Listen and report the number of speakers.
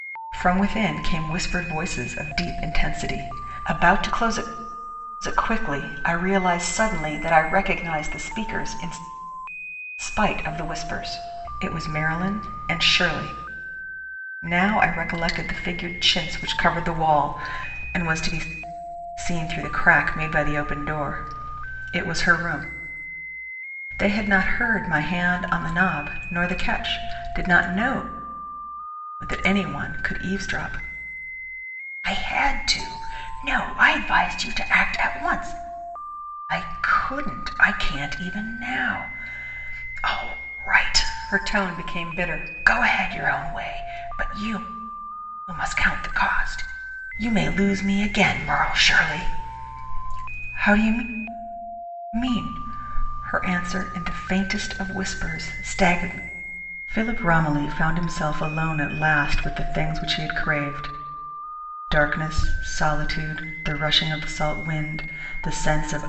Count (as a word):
one